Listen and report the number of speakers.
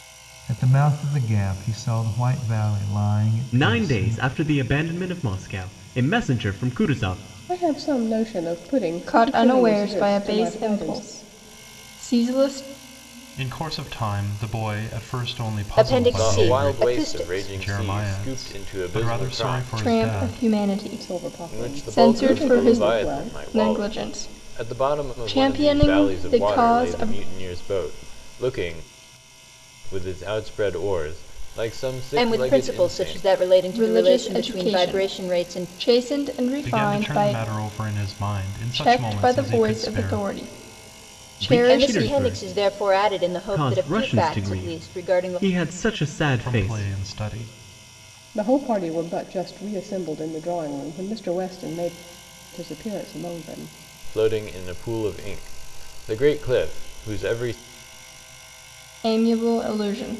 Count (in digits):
7